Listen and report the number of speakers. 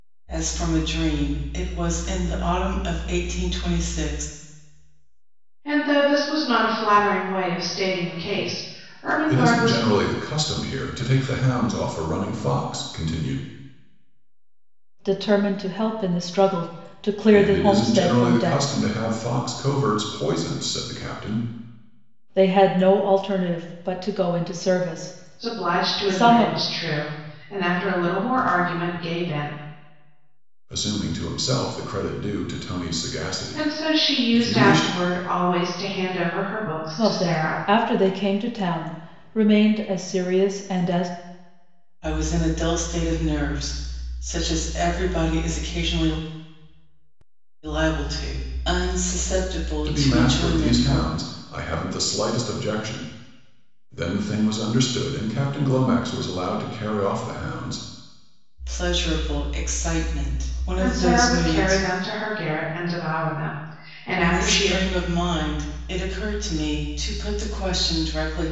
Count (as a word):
four